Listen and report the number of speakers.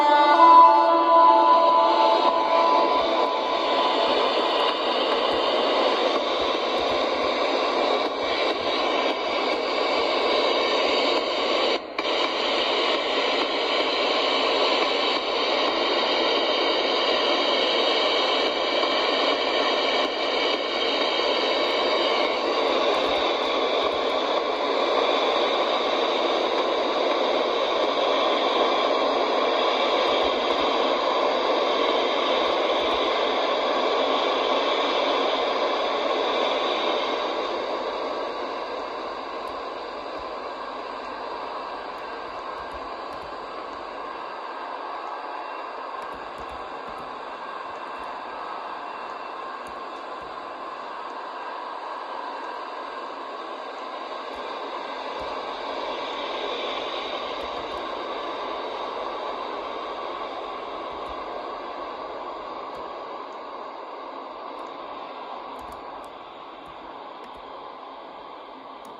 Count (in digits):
0